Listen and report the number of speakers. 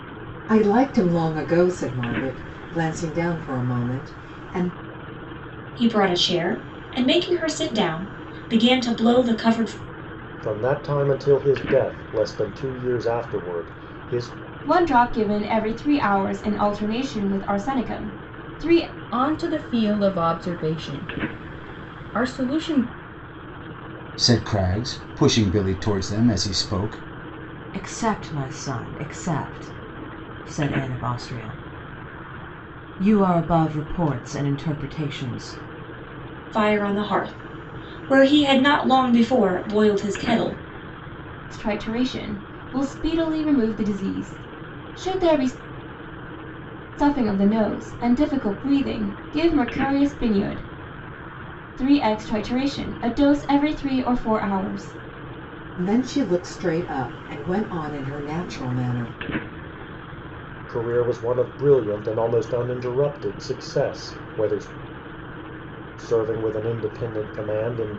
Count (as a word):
seven